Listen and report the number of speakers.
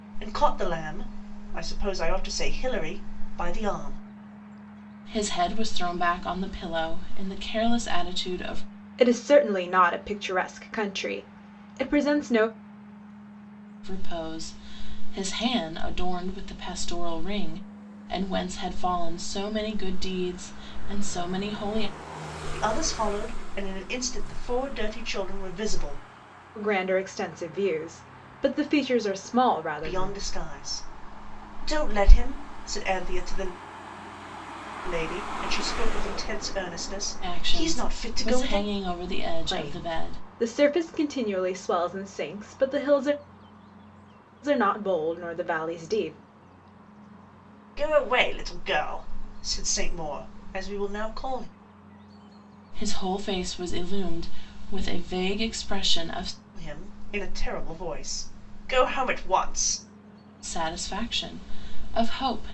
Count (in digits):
3